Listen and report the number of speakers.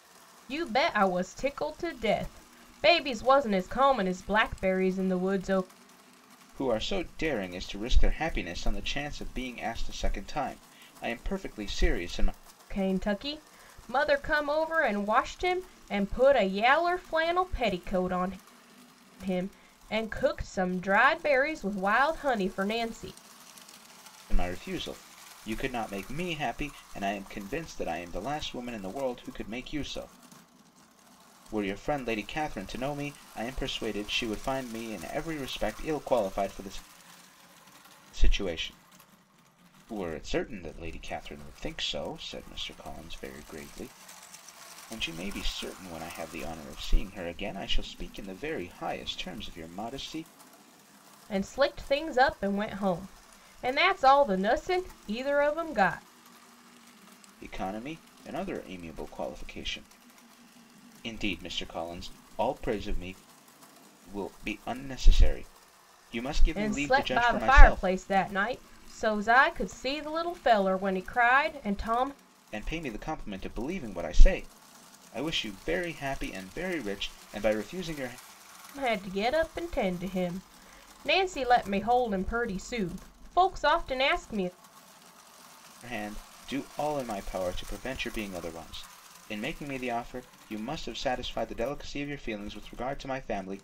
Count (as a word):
two